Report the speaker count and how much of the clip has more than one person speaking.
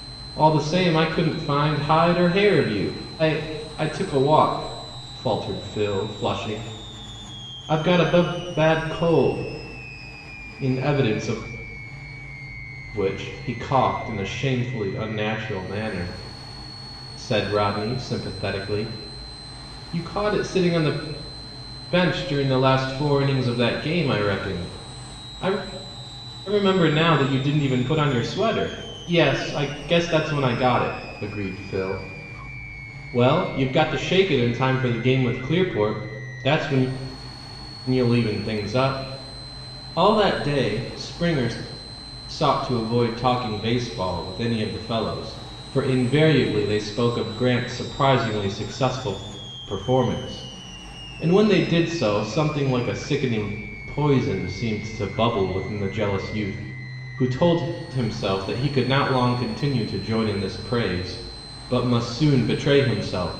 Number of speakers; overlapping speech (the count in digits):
1, no overlap